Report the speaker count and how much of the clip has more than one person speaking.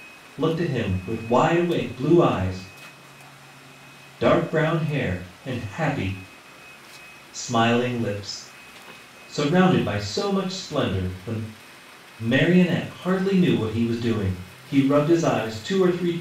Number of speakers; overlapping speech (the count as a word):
one, no overlap